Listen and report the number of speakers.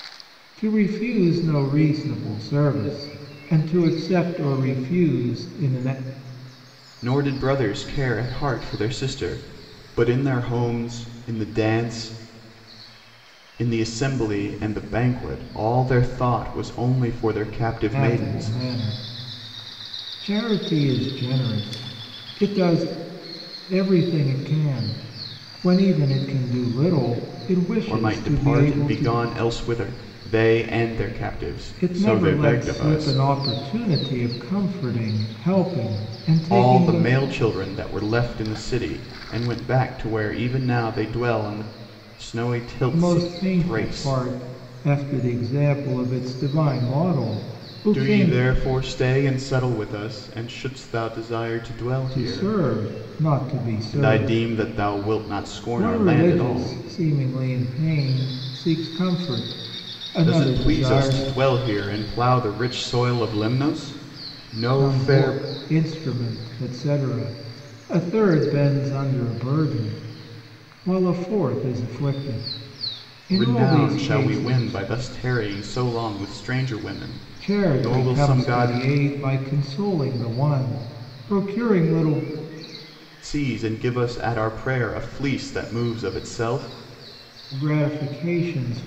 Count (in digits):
2